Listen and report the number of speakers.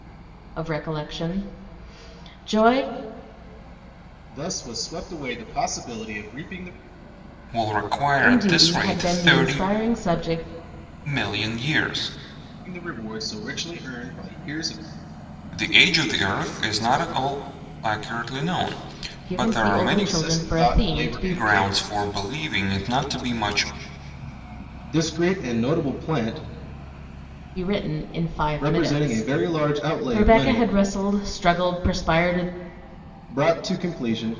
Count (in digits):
3